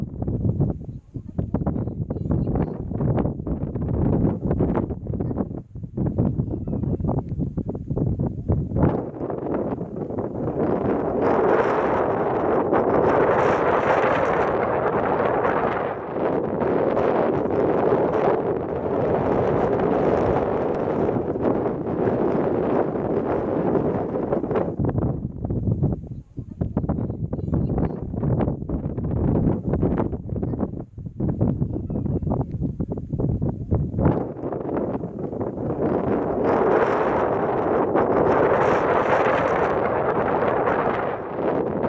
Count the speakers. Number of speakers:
zero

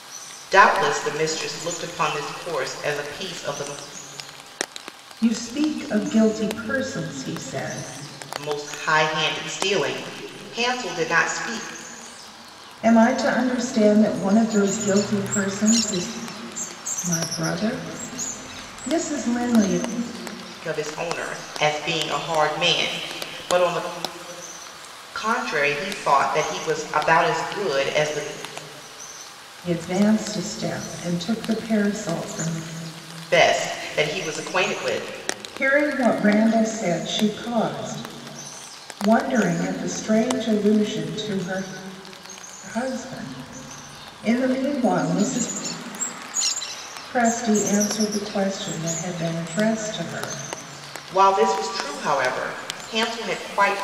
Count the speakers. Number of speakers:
two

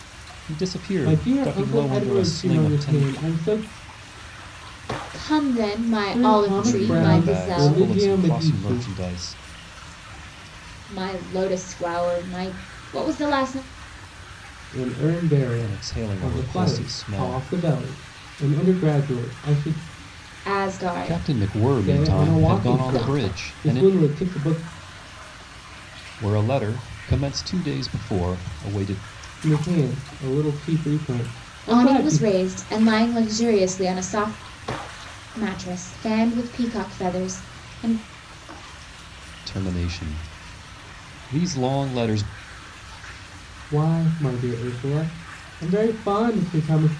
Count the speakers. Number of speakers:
three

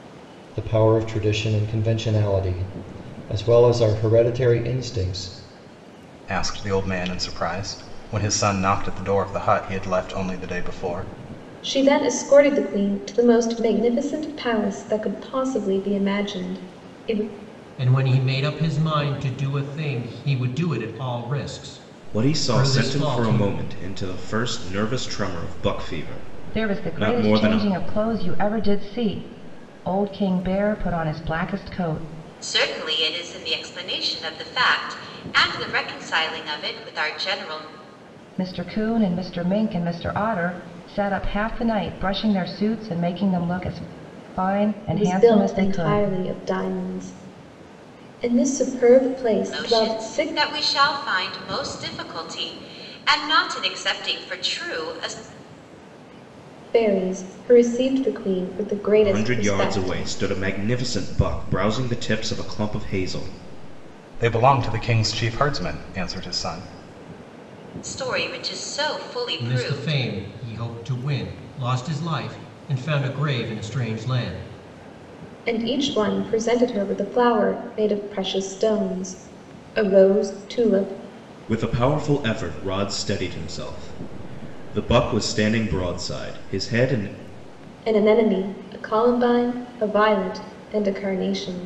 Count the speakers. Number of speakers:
seven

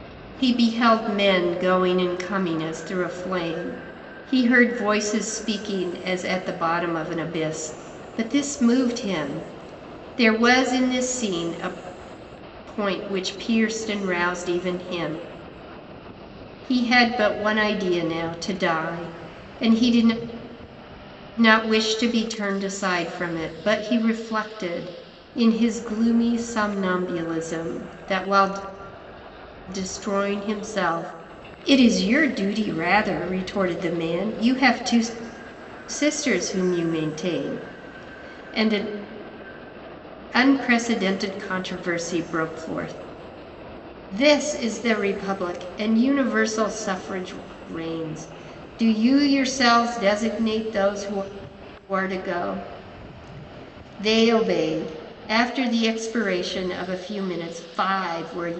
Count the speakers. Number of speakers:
one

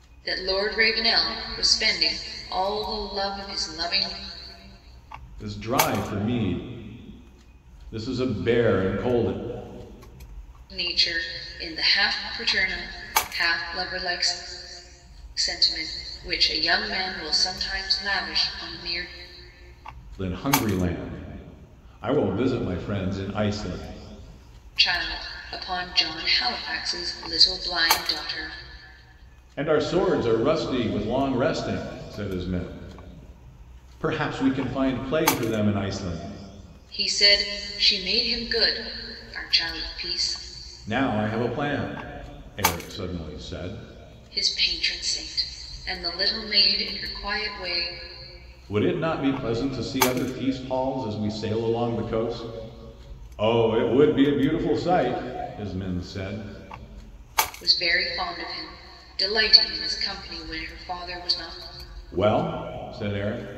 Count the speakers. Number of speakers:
two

